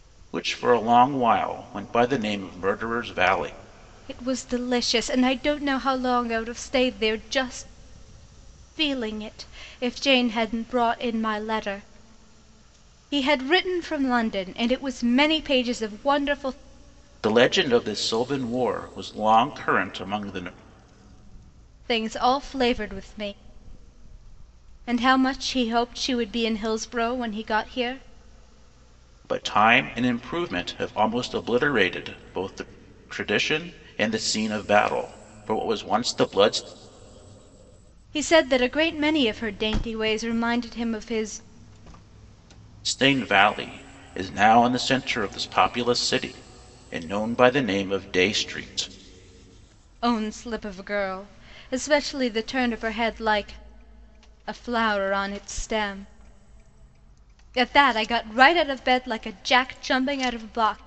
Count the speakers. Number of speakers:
2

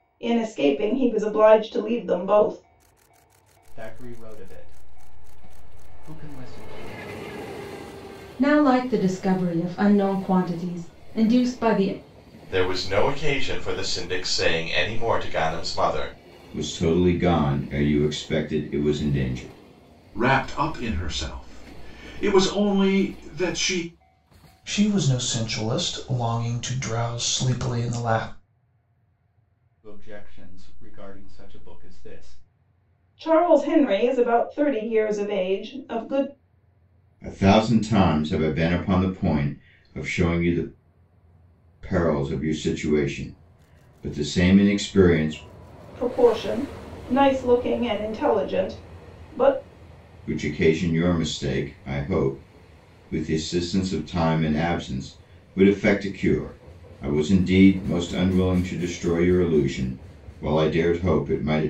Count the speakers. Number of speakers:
7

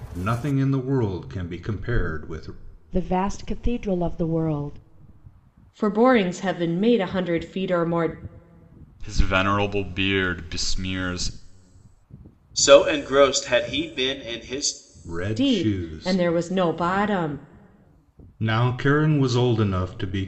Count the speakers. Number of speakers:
5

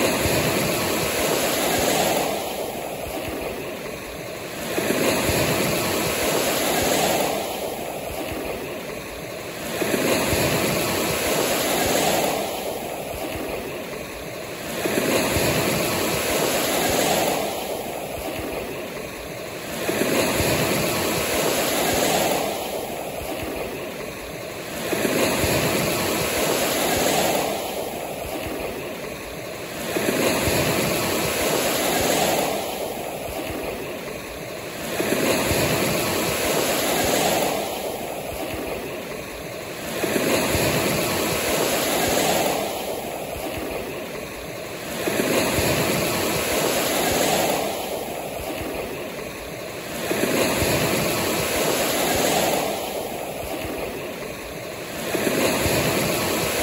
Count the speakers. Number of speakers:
0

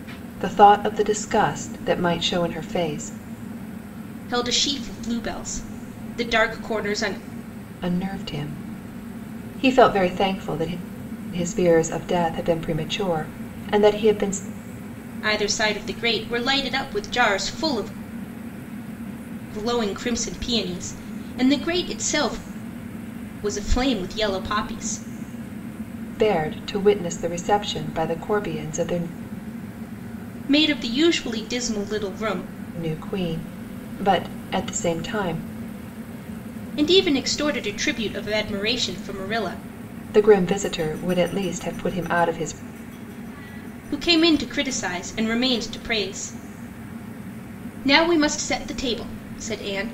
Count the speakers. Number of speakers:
2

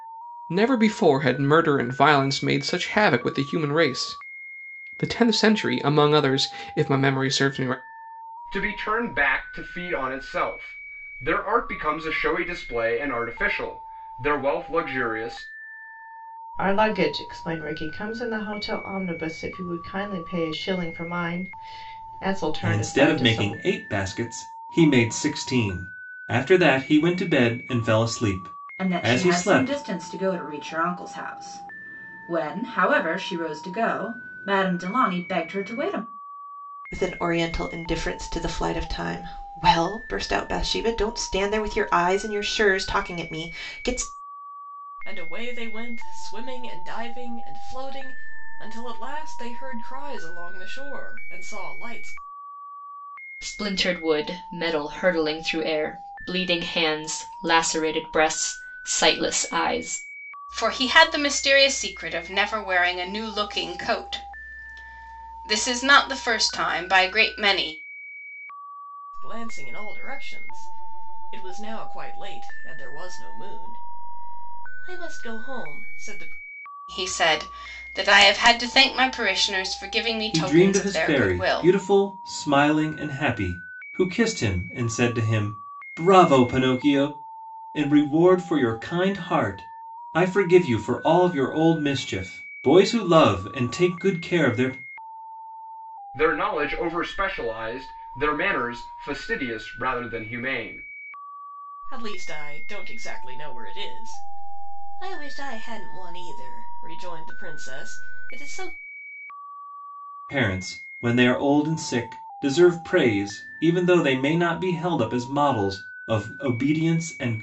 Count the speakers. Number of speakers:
9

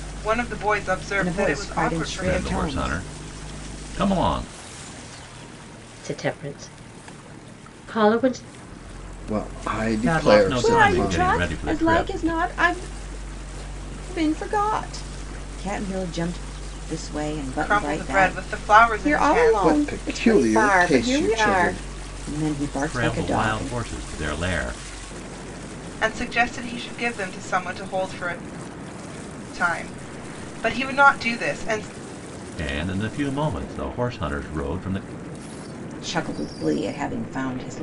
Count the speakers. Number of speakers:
5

